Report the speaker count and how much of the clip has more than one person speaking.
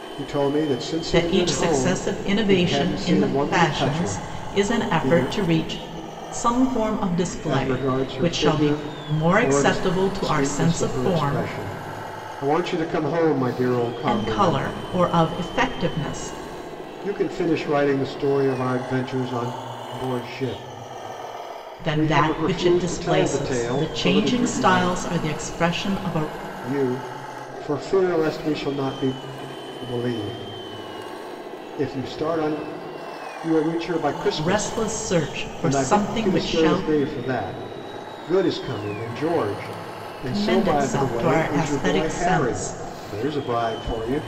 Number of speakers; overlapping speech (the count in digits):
2, about 37%